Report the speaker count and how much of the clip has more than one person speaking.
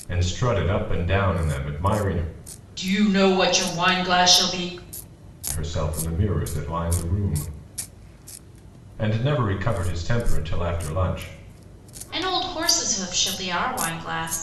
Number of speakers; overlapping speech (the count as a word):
two, no overlap